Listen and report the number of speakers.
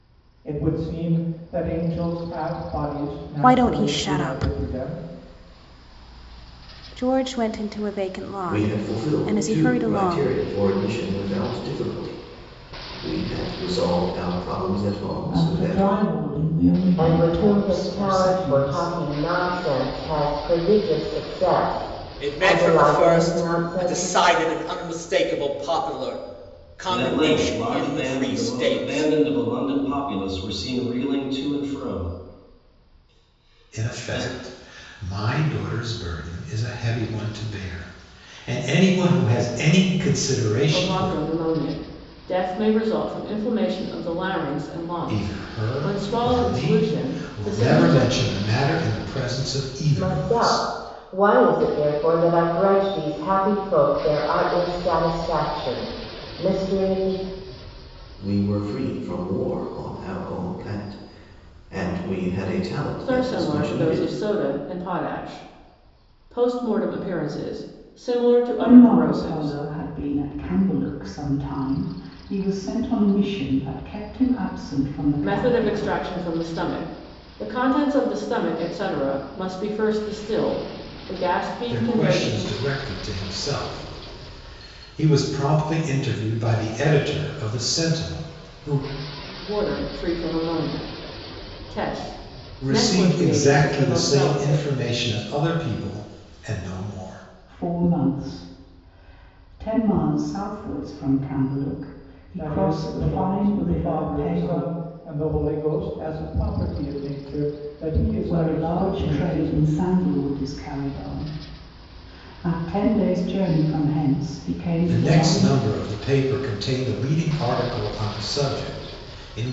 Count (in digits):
9